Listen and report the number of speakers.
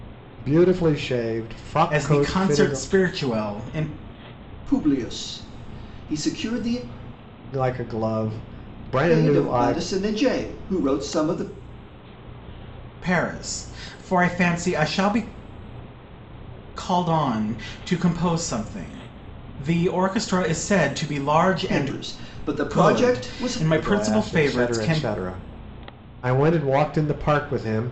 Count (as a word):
three